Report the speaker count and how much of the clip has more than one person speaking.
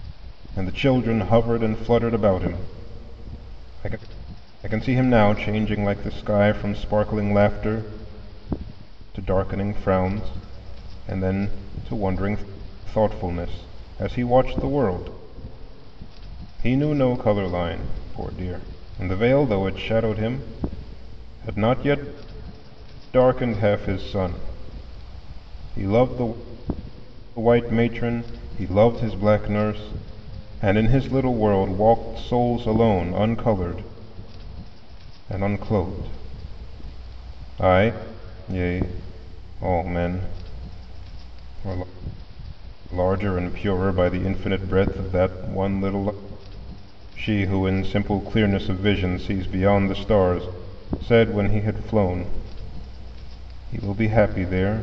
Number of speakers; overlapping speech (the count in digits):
1, no overlap